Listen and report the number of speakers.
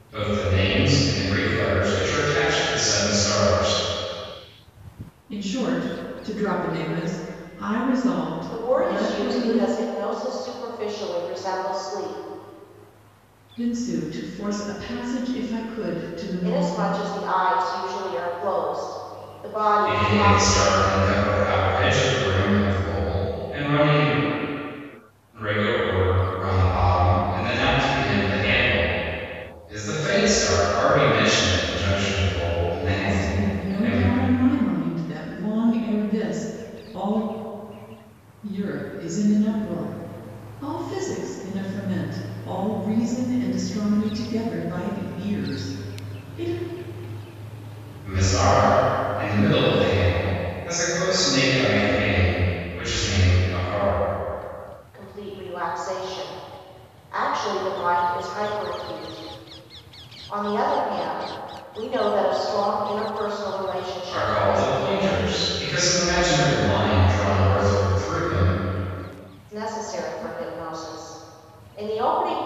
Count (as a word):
three